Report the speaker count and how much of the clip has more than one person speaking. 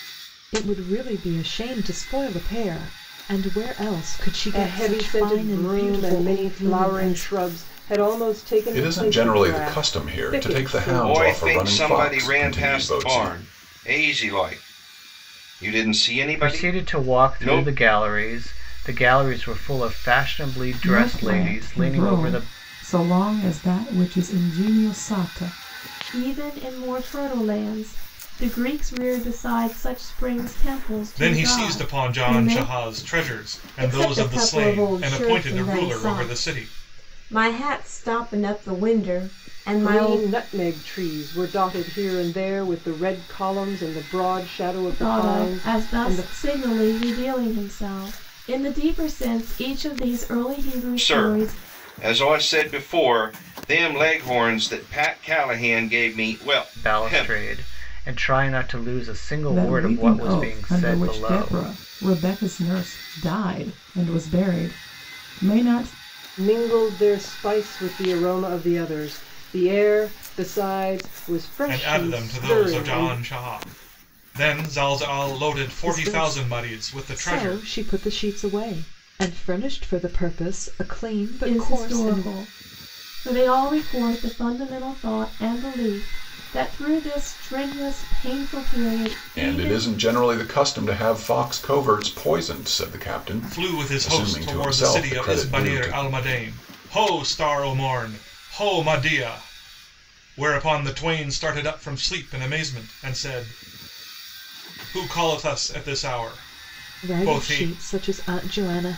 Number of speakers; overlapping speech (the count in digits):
9, about 26%